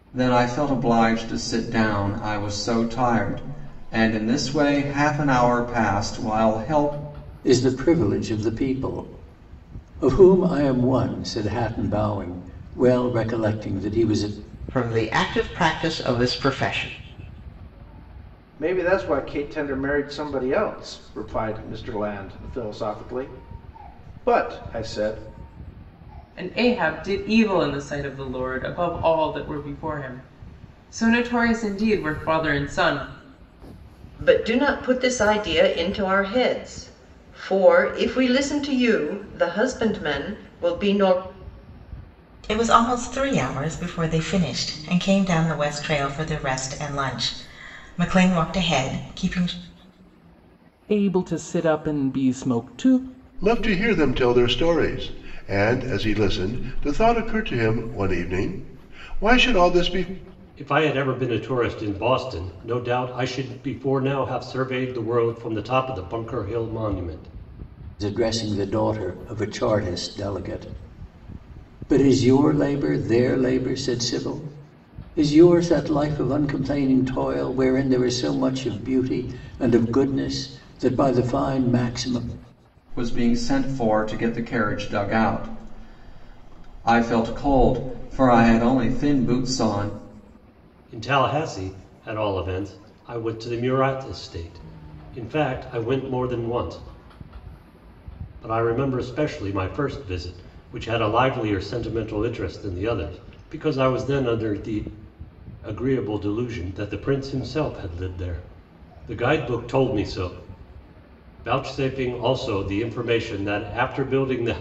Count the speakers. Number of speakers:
ten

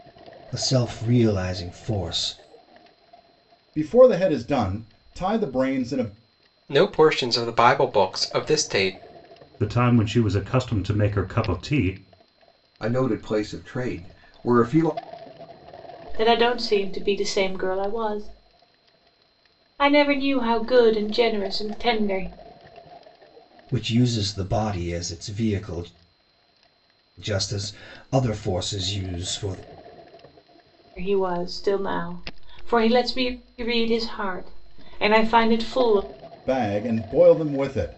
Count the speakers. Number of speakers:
six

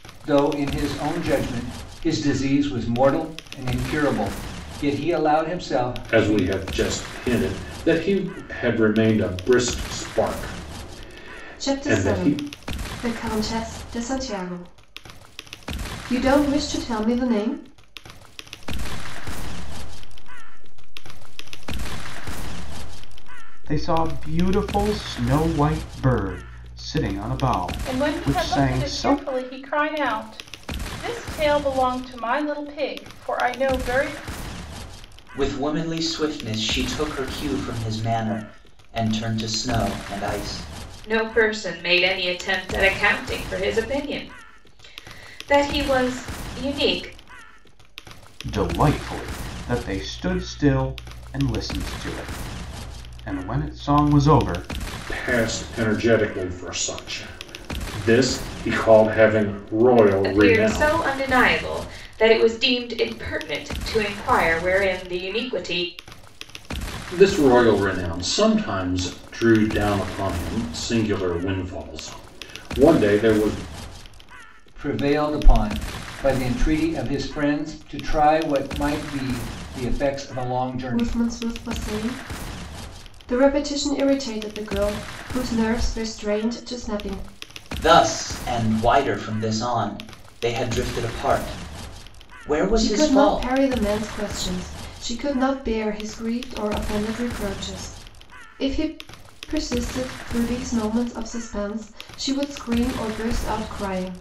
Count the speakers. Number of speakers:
eight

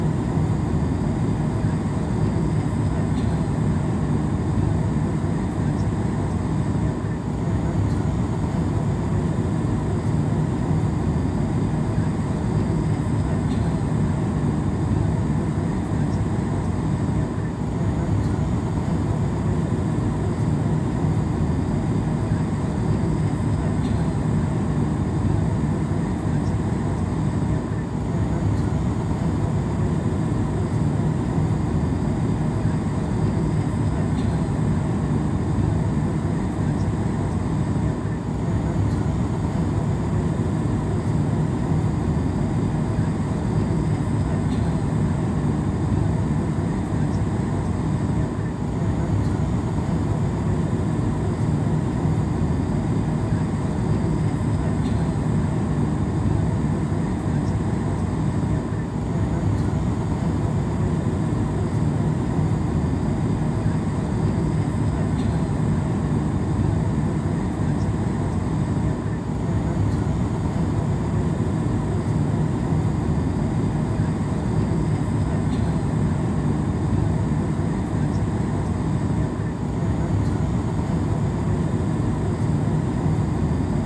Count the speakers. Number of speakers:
zero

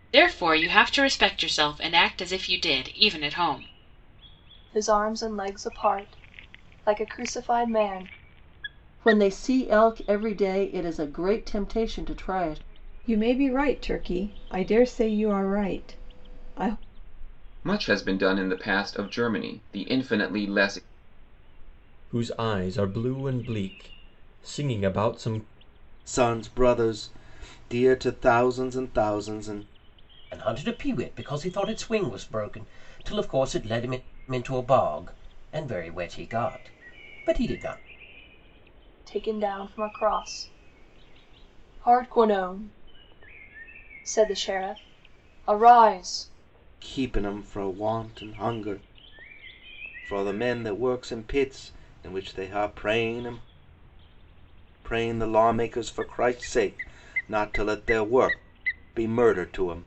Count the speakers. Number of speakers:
eight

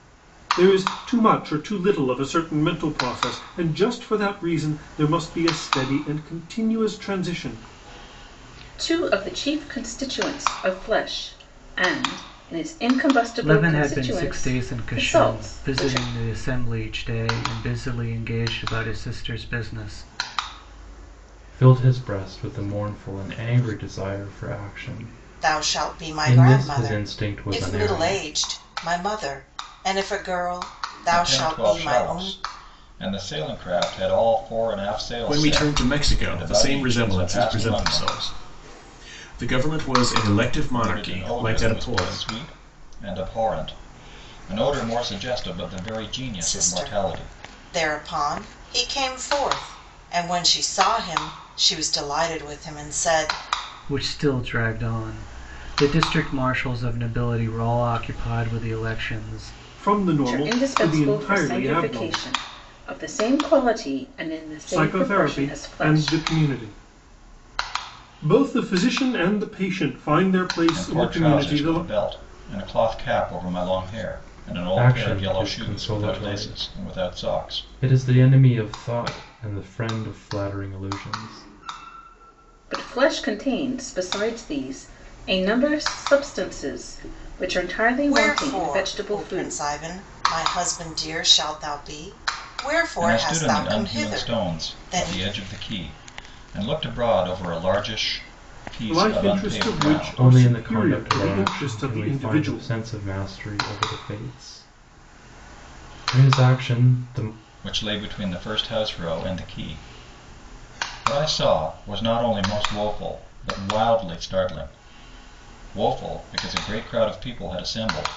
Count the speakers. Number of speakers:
seven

